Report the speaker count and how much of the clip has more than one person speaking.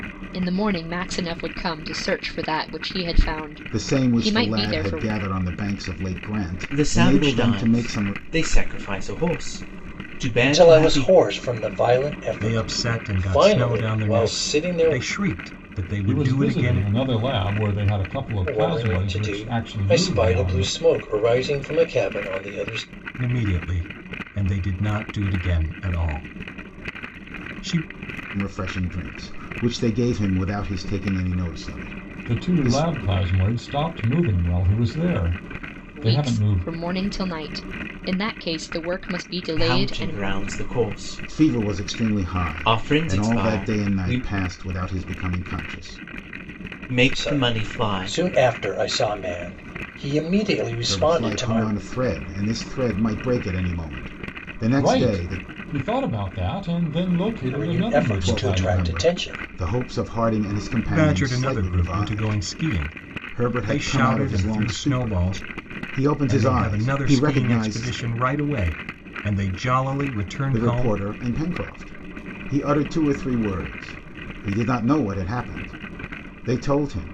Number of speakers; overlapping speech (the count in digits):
6, about 32%